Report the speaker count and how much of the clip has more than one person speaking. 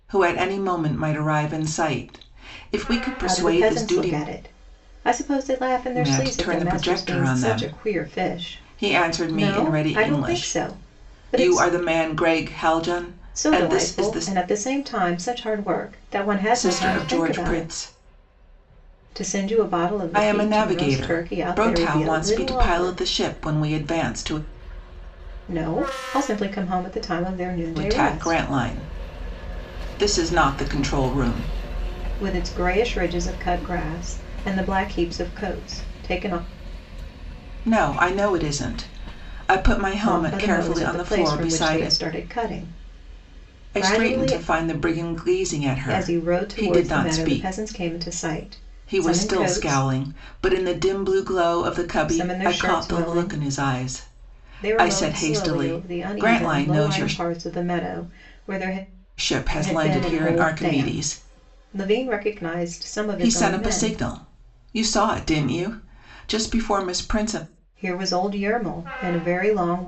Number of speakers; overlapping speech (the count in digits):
2, about 34%